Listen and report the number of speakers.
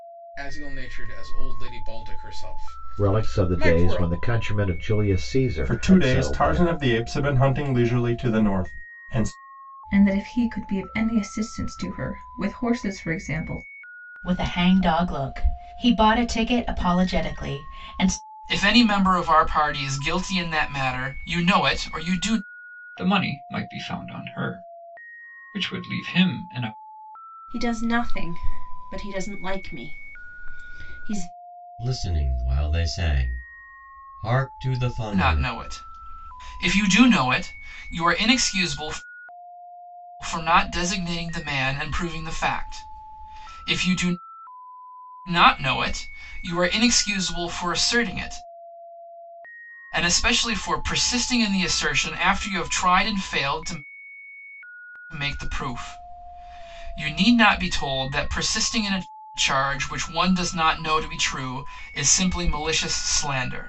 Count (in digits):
9